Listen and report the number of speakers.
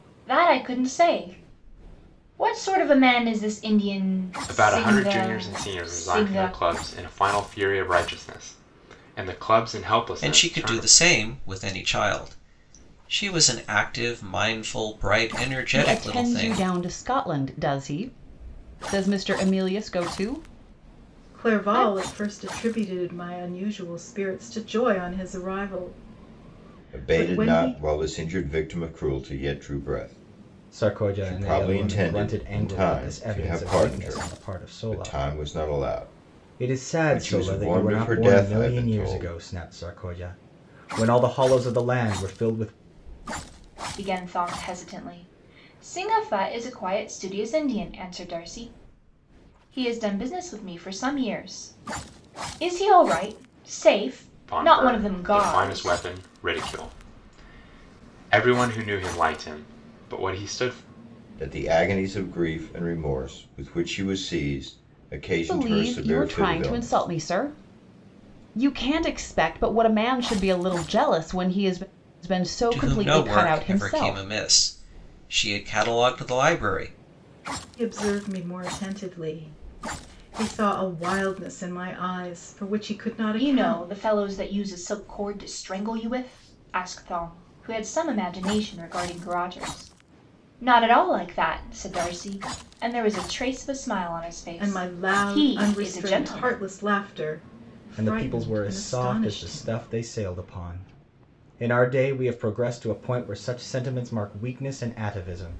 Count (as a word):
seven